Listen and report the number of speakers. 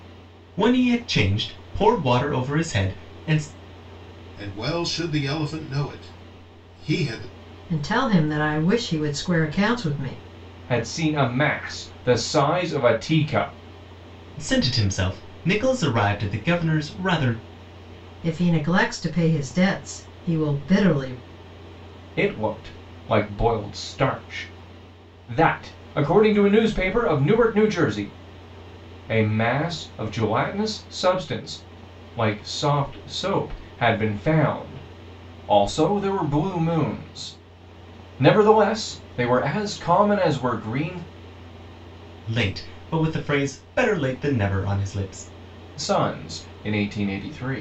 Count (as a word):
four